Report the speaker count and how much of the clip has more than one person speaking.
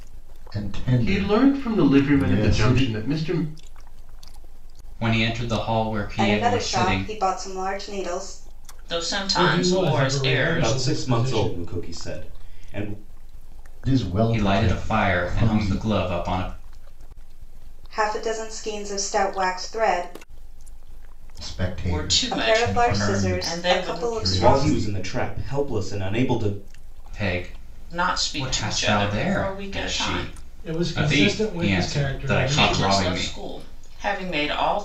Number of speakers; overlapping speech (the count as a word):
seven, about 43%